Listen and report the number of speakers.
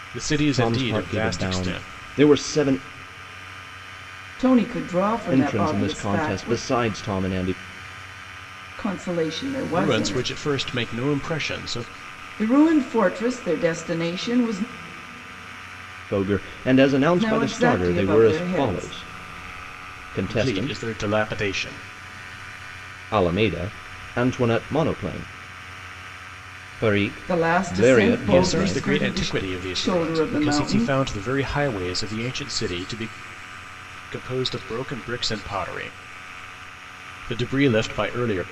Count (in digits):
3